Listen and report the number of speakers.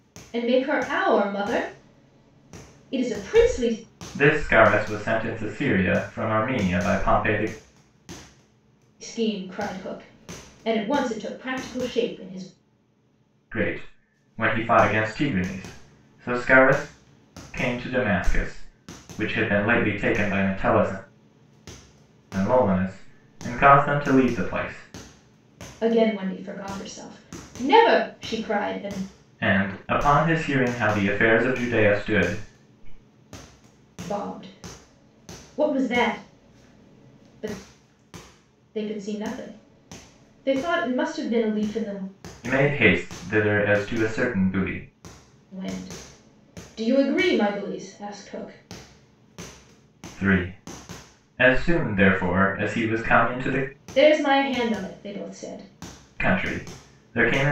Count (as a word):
two